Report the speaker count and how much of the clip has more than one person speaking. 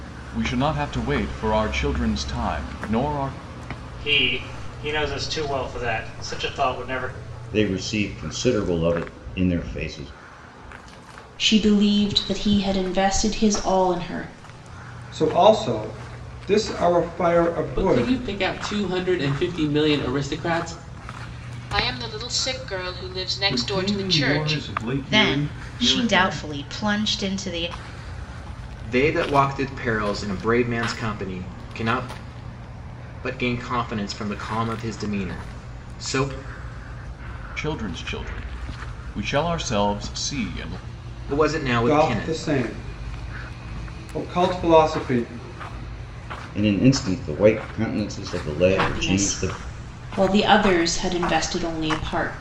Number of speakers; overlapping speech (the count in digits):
10, about 9%